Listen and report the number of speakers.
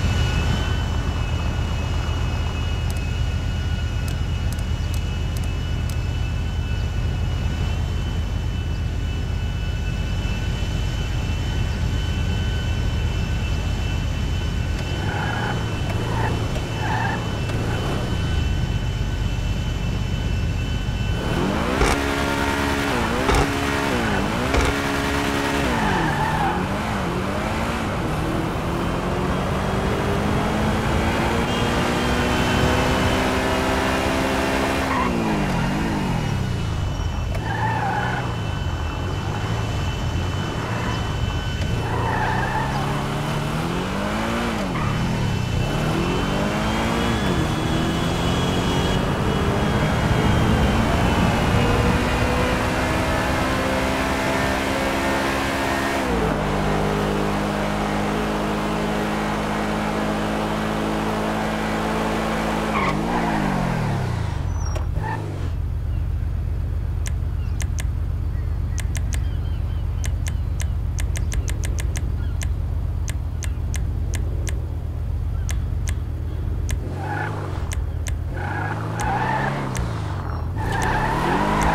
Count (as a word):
zero